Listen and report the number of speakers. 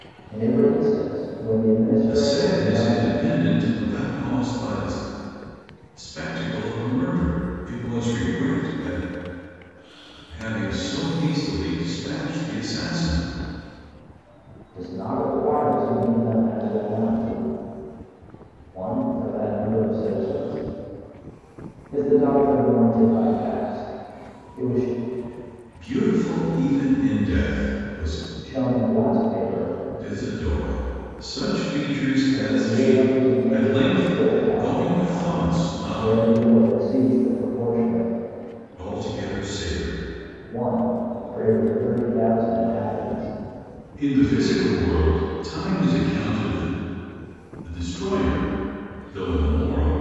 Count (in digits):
2